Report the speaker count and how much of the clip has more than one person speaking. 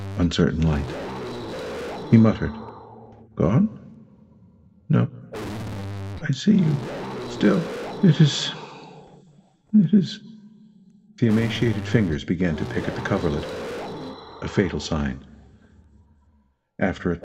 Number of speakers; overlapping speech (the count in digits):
1, no overlap